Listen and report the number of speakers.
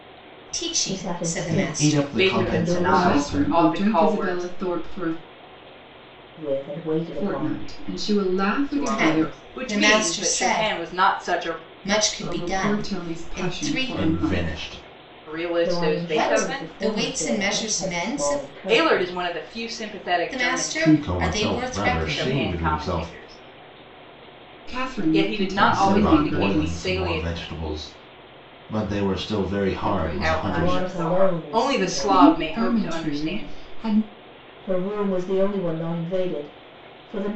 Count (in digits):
5